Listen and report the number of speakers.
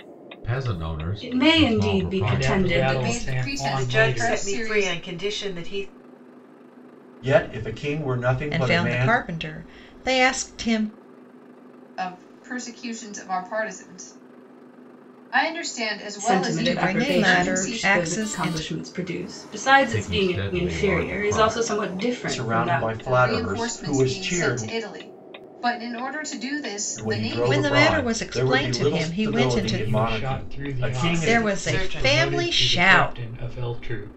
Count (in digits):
7